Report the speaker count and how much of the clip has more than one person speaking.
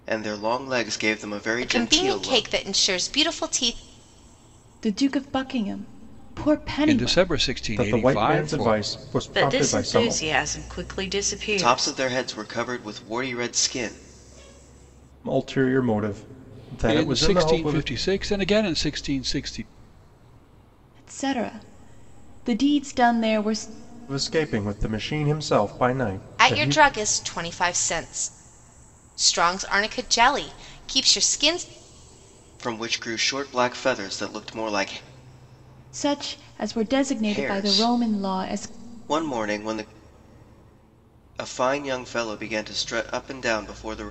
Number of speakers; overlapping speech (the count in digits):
6, about 16%